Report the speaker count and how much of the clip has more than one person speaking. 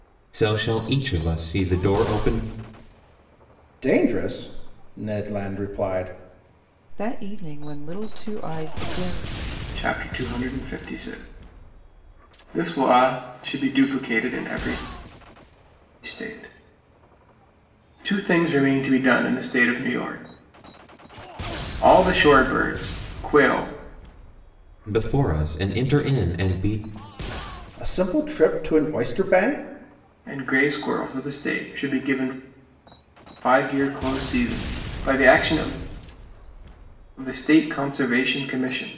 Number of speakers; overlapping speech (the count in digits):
4, no overlap